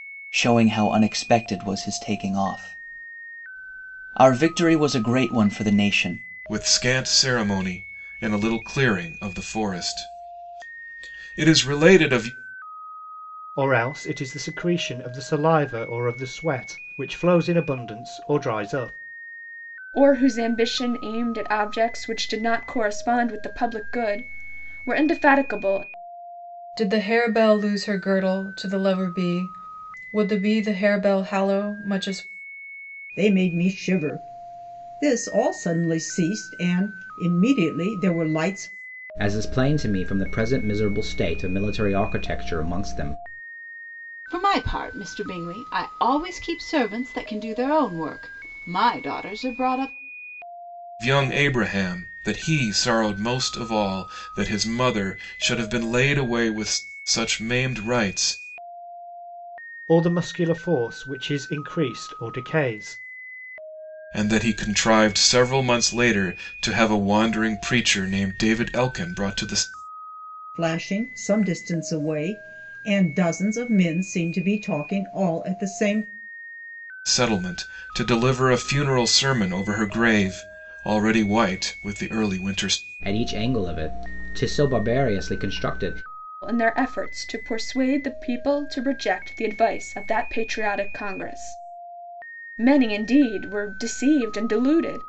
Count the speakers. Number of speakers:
eight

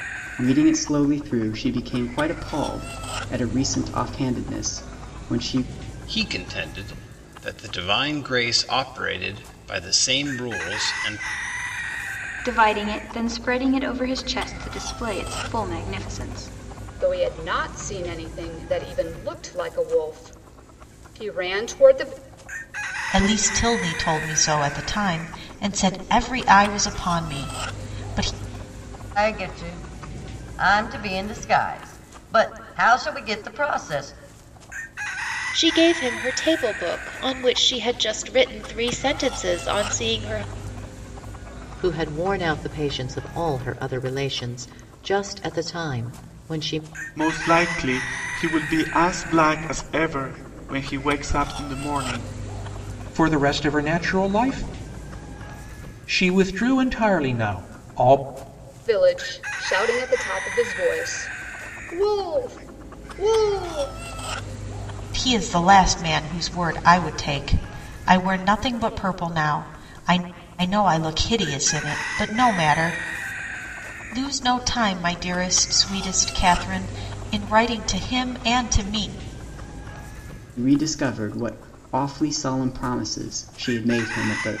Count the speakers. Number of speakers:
ten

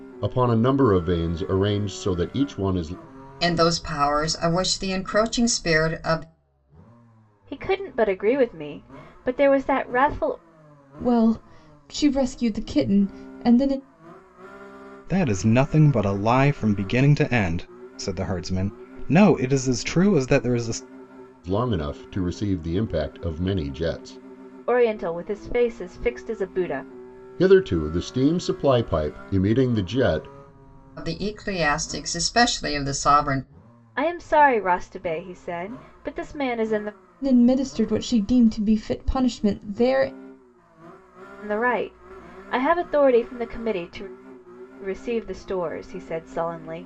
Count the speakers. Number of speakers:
five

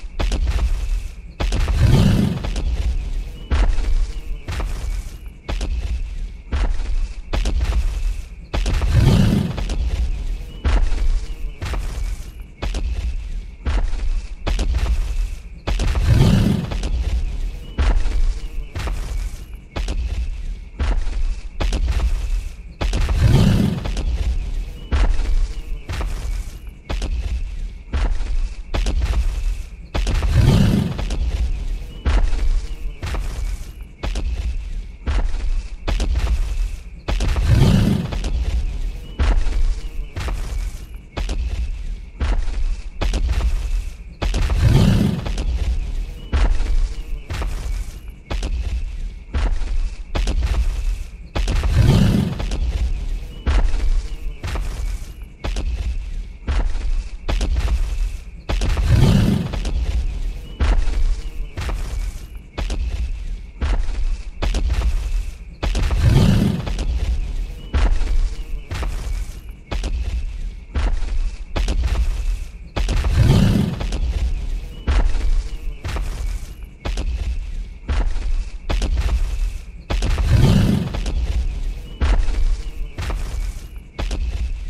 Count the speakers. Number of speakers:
zero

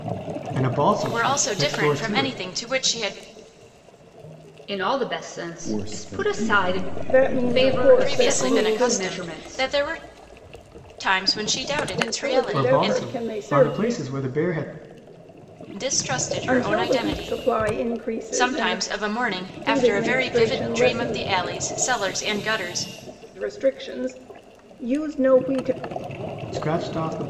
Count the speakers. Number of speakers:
five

